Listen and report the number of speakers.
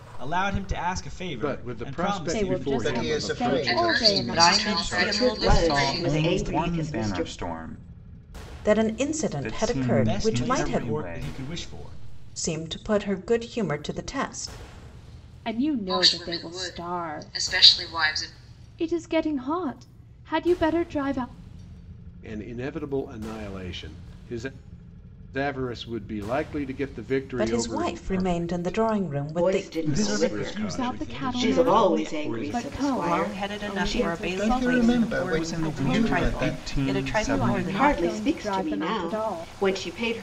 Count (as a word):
nine